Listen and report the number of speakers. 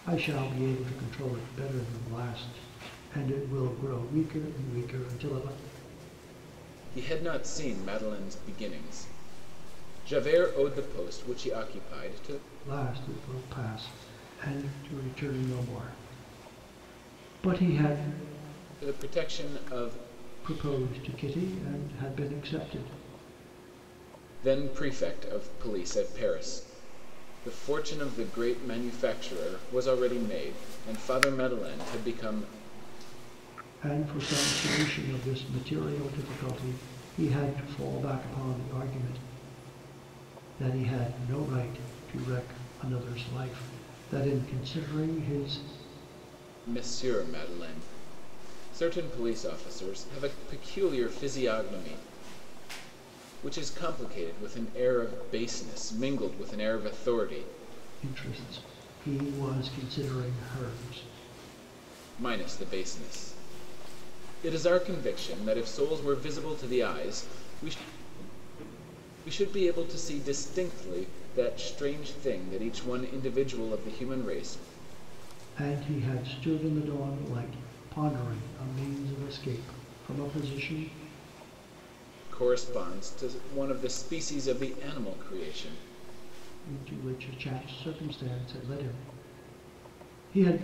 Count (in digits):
2